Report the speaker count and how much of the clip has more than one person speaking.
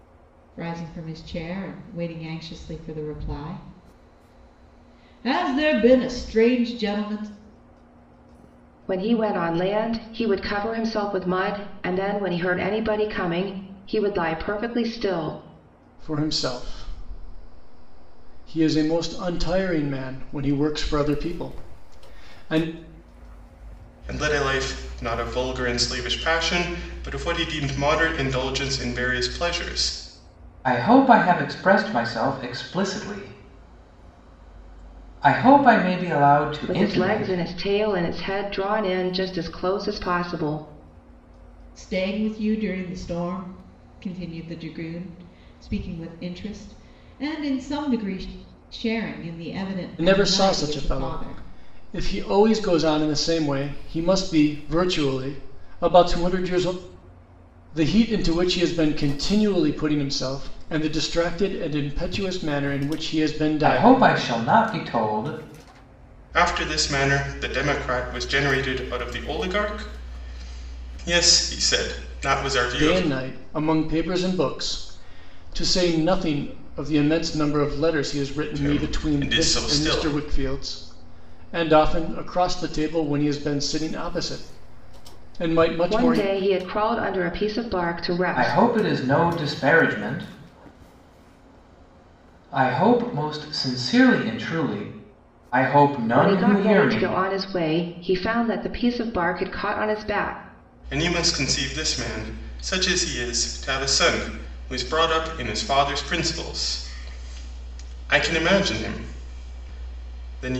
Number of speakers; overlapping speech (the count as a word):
five, about 6%